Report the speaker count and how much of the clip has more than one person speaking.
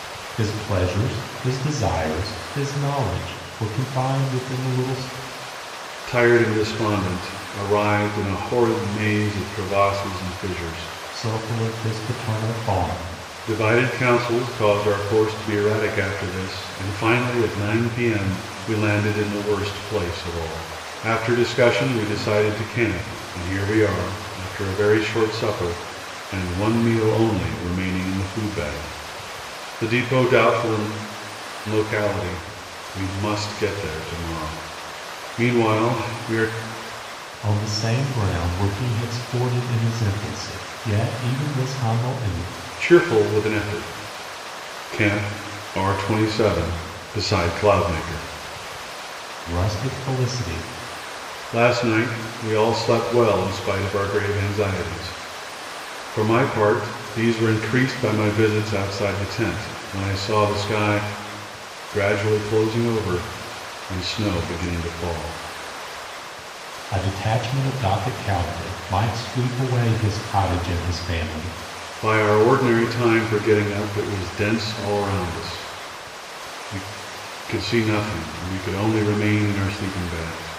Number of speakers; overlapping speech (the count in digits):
2, no overlap